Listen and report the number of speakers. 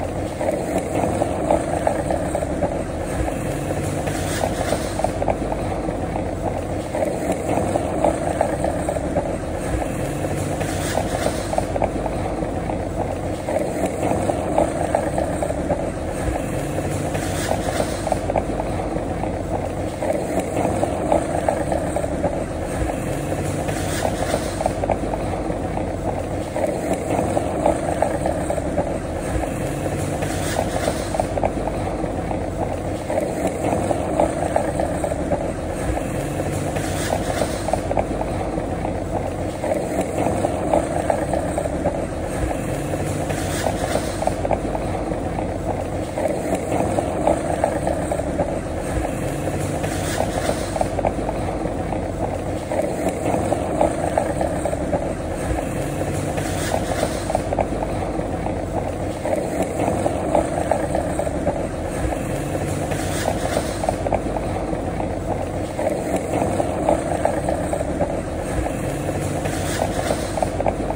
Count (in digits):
0